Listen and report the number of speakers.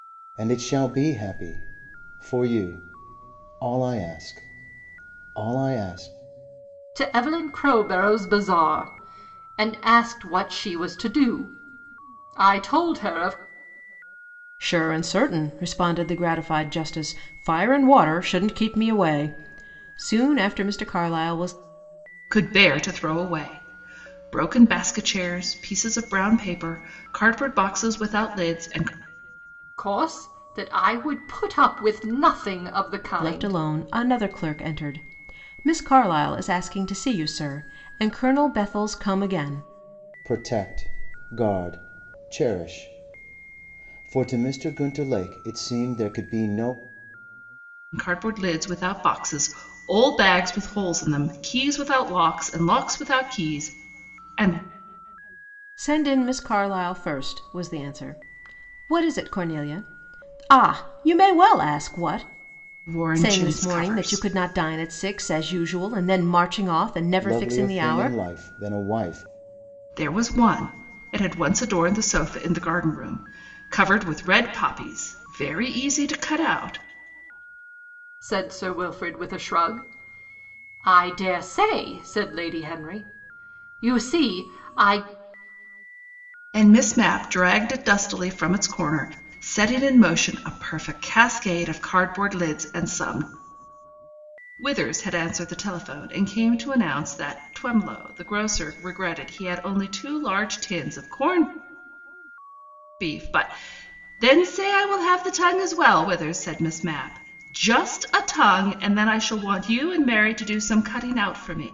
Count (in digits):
4